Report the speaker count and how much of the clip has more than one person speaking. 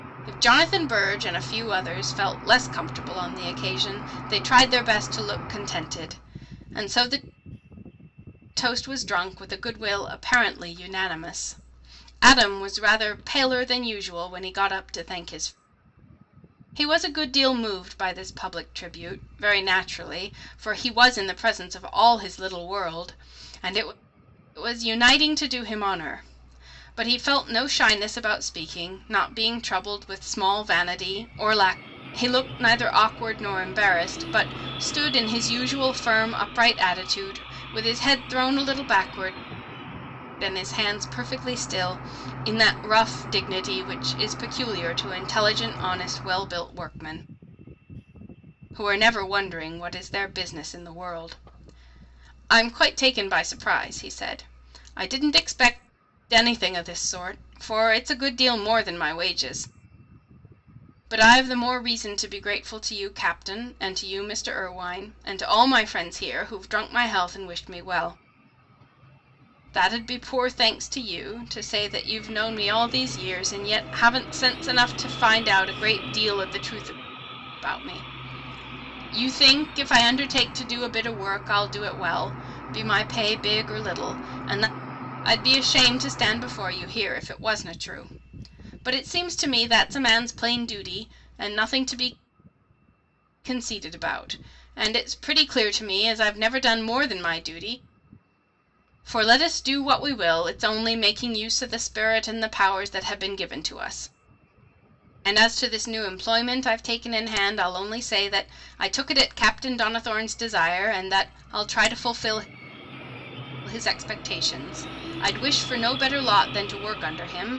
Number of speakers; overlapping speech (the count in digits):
1, no overlap